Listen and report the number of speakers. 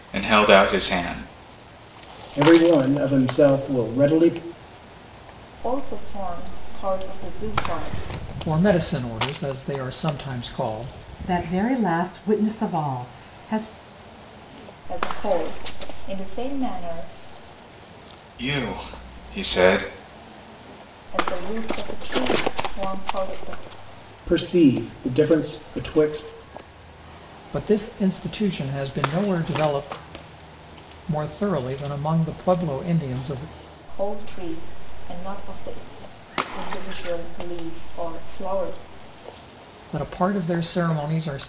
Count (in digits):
5